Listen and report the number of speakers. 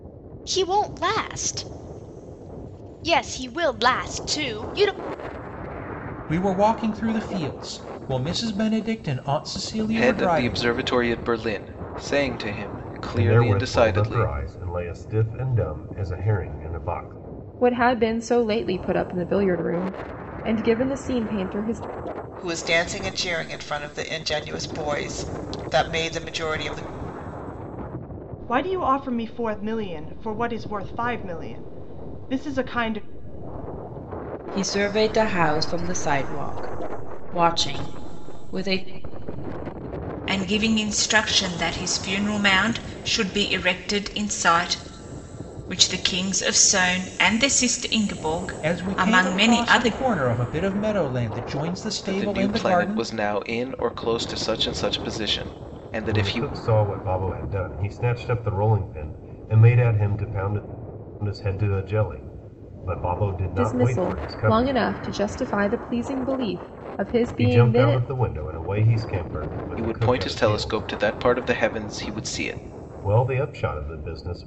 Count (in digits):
9